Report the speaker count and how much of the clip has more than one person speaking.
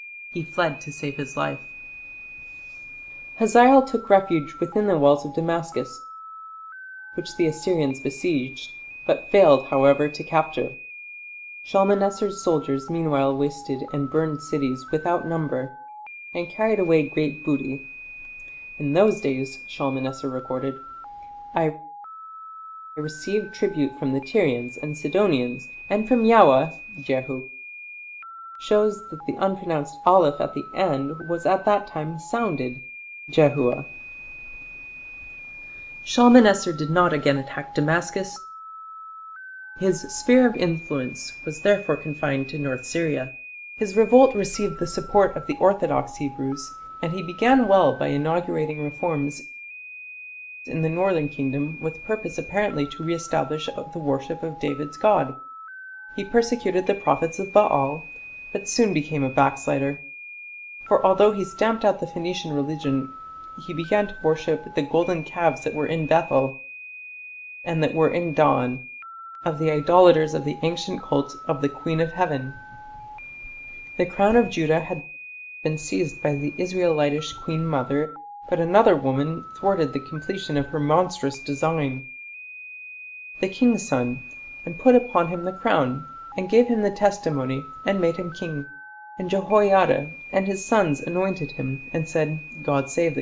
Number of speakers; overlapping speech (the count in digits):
1, no overlap